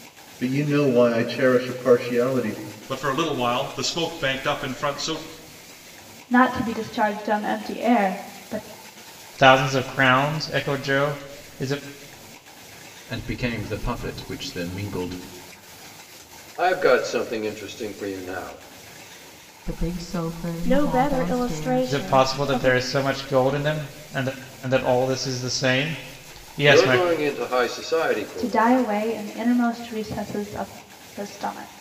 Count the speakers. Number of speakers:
8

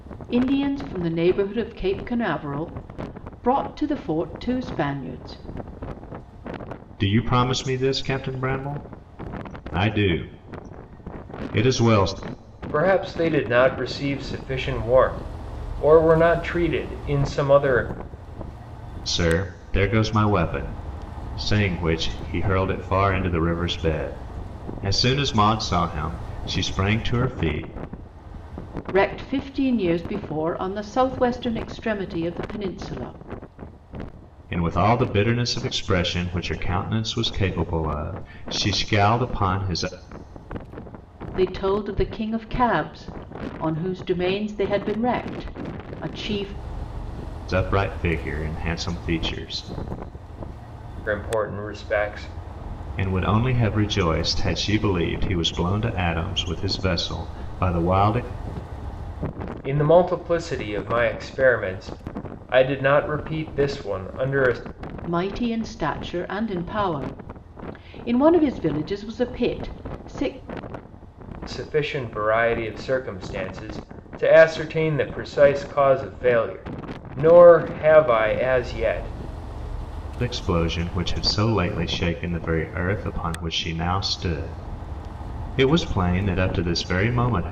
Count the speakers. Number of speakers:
3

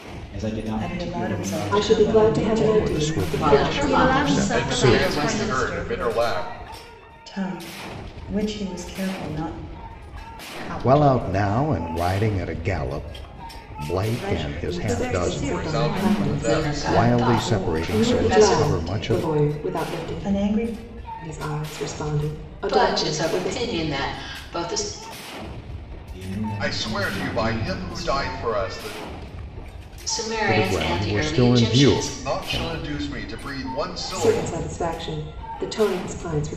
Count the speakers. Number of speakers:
8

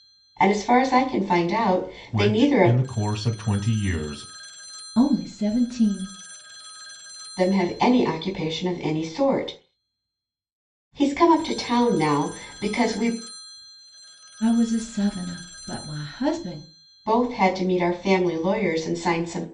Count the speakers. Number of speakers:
3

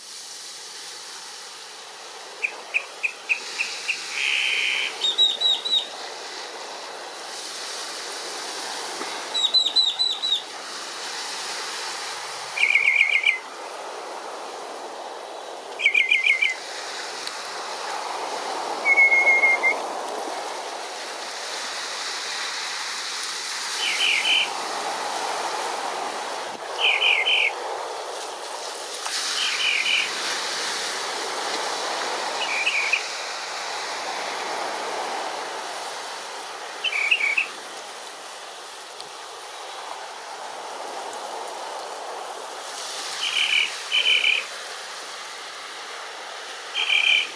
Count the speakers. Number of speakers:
0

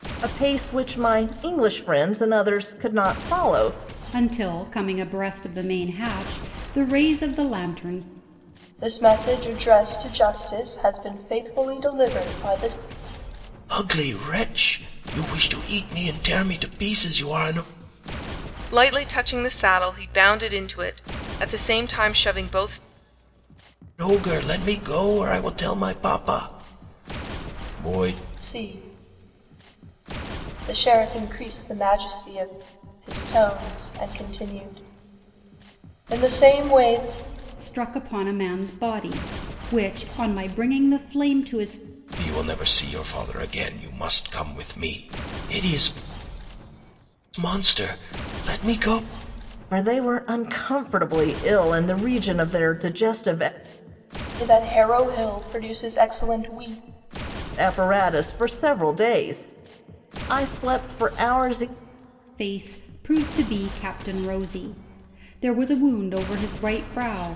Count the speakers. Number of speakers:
5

